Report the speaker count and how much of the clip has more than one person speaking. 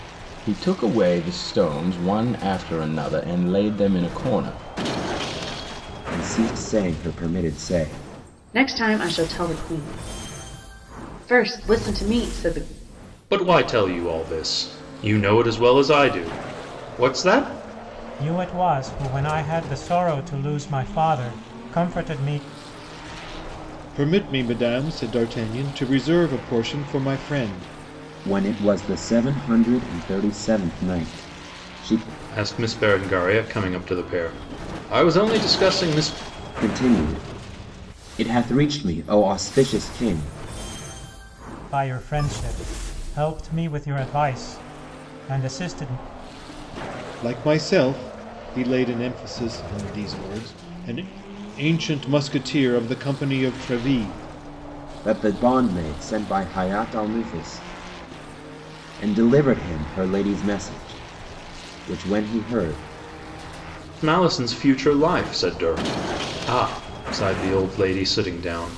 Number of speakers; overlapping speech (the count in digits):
6, no overlap